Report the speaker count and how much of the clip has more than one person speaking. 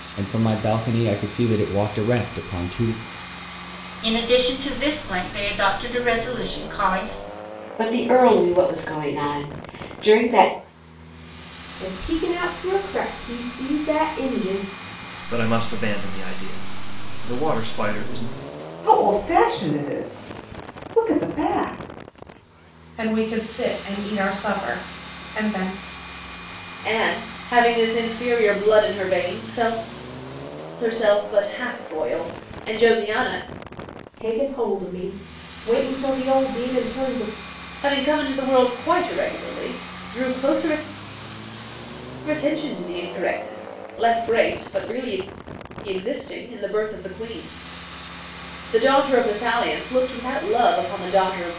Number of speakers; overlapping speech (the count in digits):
8, no overlap